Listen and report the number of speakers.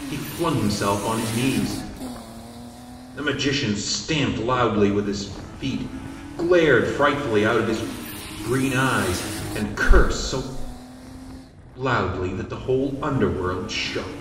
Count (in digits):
1